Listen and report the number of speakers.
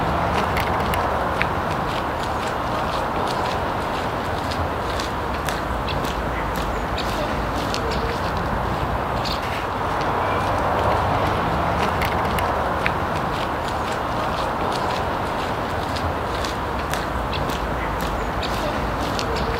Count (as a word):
zero